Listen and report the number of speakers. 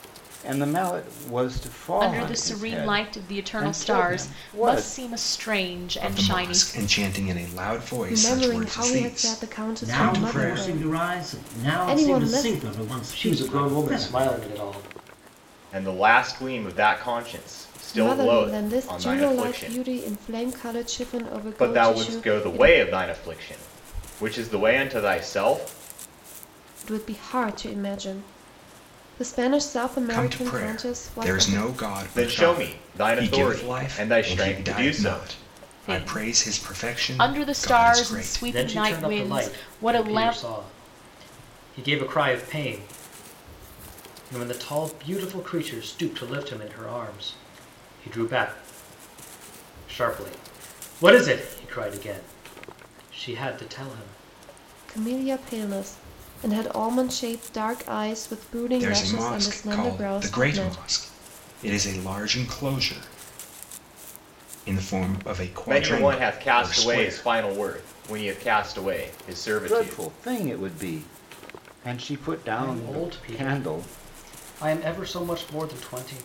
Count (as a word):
seven